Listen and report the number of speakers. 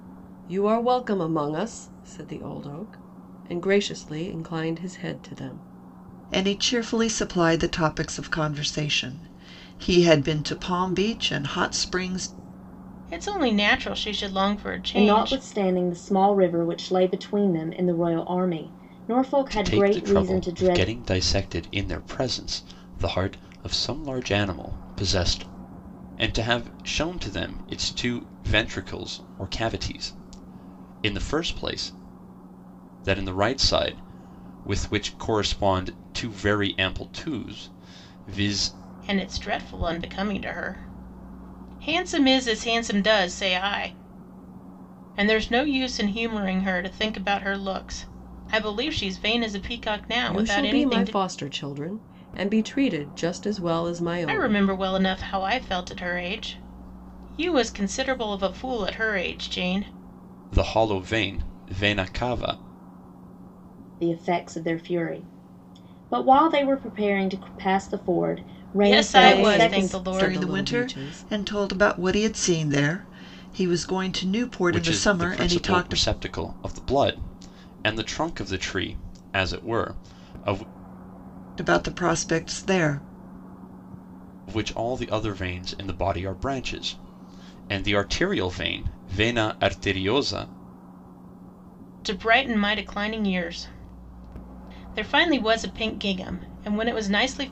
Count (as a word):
five